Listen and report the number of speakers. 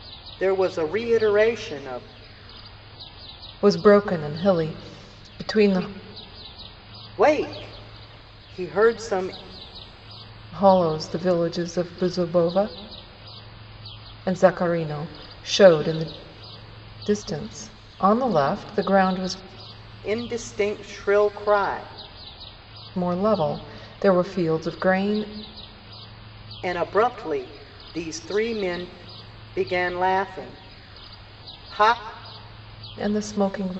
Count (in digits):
2